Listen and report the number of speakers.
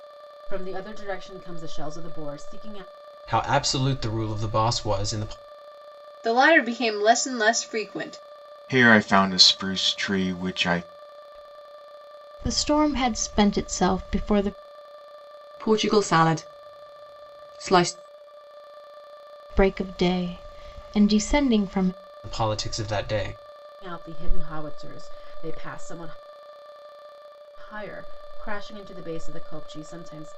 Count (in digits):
6